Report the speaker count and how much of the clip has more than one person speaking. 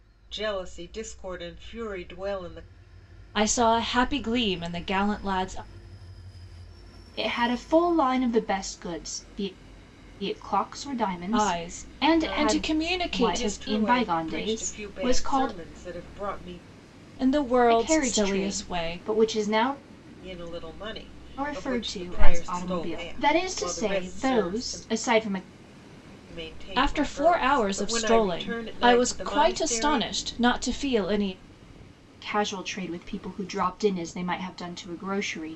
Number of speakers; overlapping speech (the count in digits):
3, about 35%